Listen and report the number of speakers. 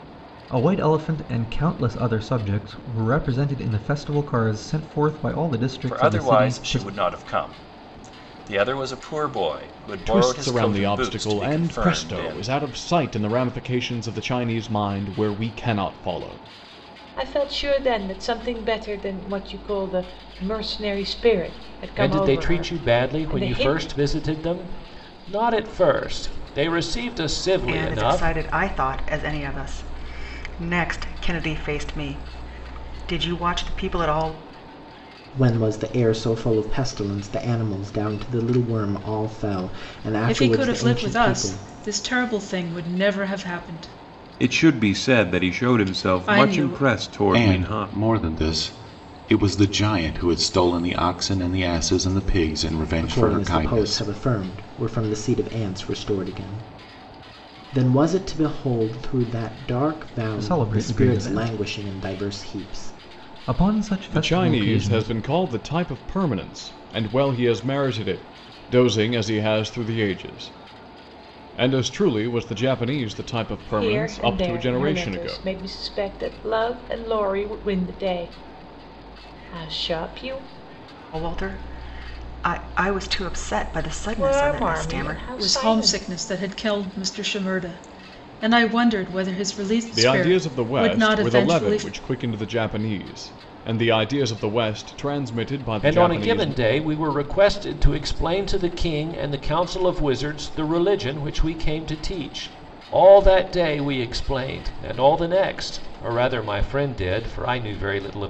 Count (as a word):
ten